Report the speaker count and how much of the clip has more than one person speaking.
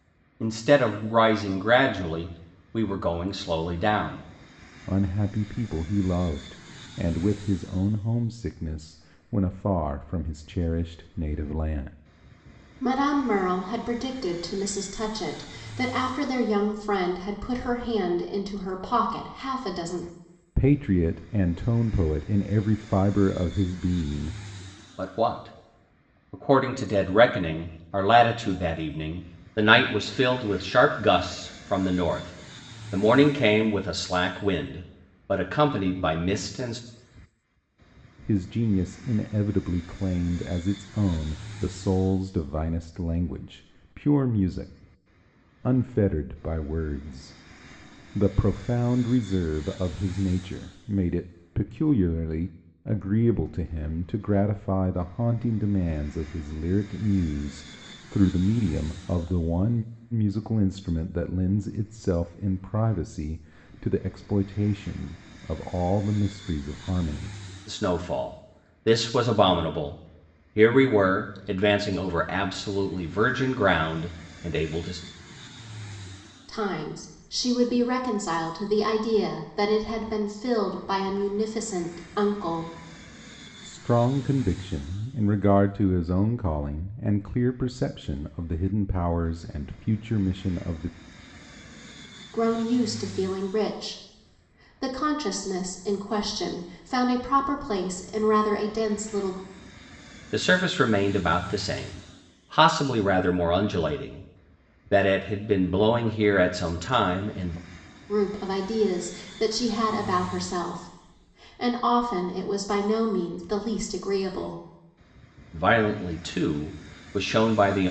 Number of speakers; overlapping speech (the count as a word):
three, no overlap